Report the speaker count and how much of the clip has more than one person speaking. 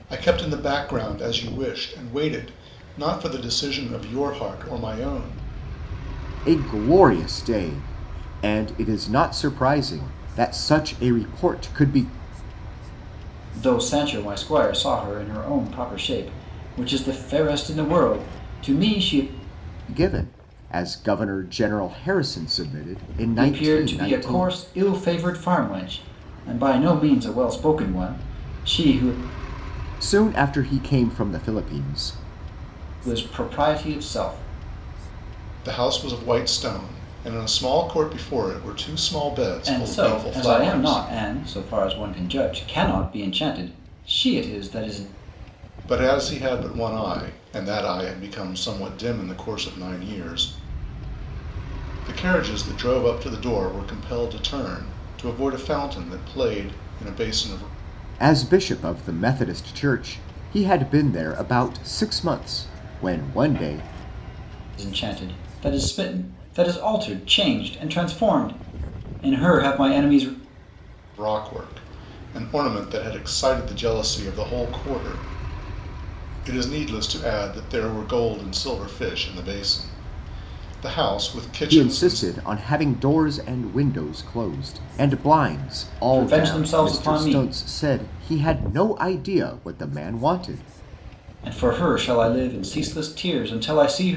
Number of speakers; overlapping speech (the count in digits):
3, about 5%